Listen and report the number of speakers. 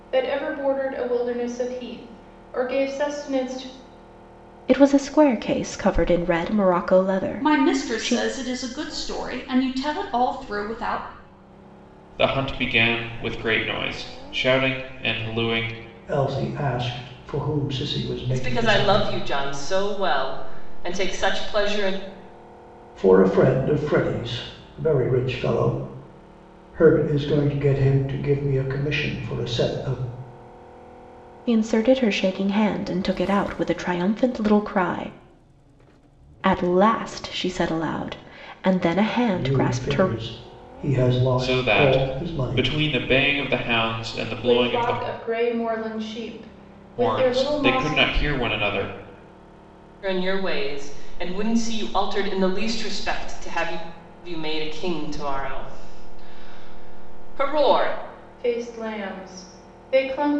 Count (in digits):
6